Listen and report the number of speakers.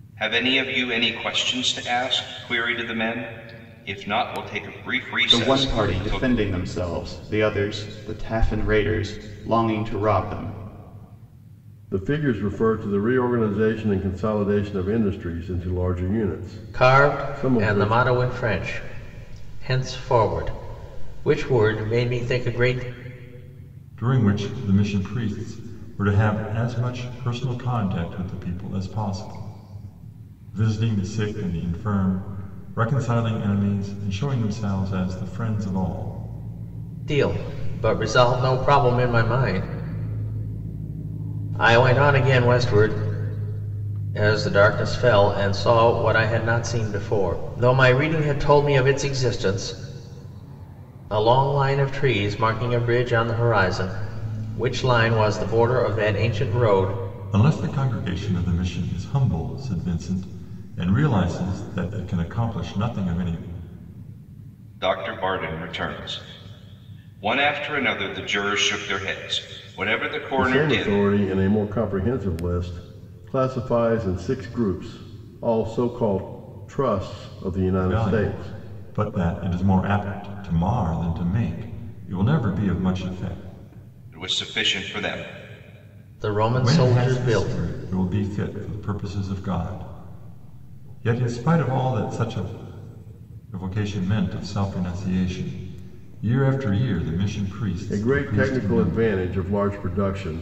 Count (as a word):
five